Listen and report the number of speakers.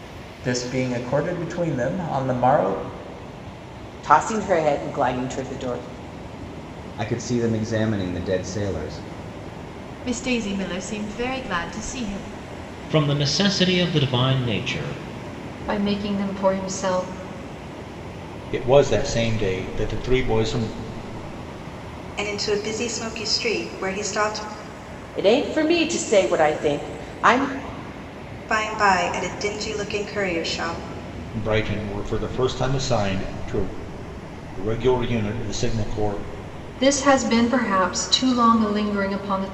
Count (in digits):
8